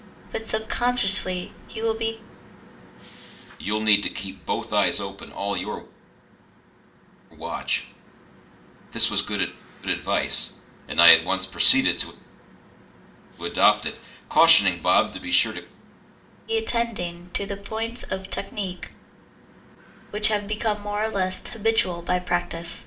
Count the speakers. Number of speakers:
2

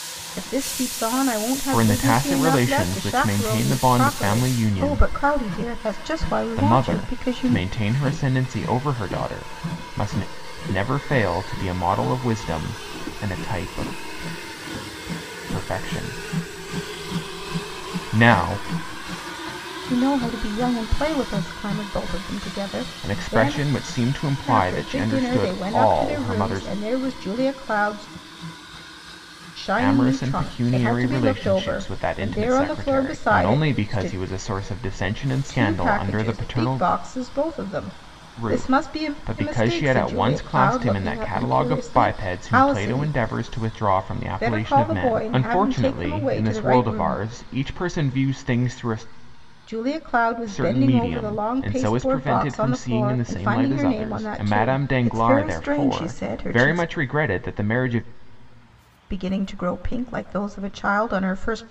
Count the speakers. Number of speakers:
2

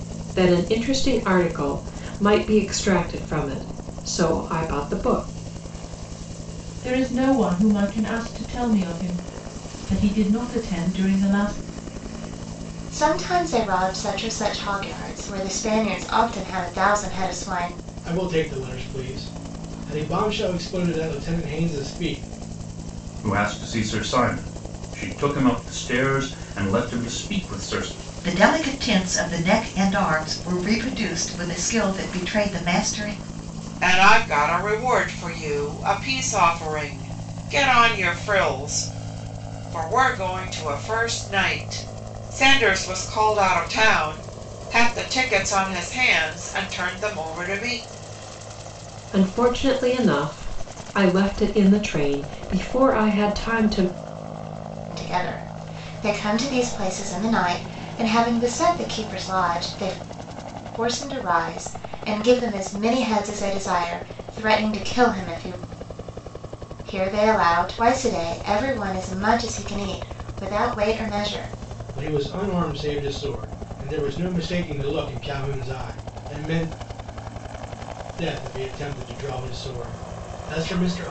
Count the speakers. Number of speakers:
7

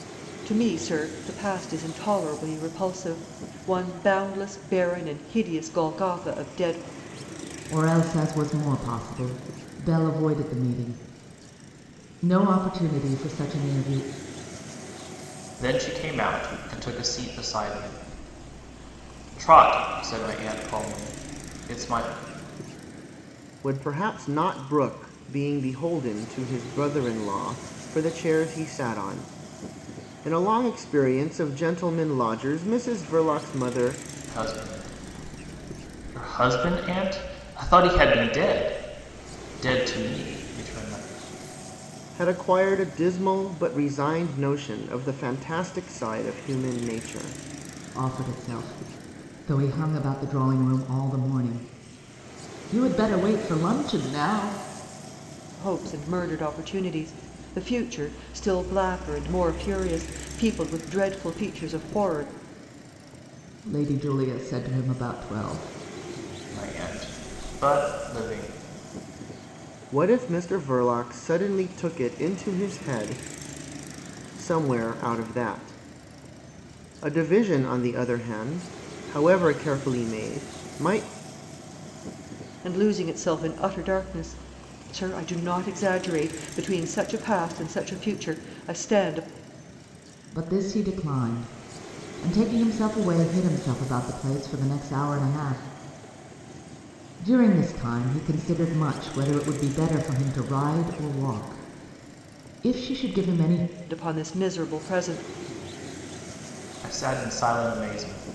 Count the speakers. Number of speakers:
4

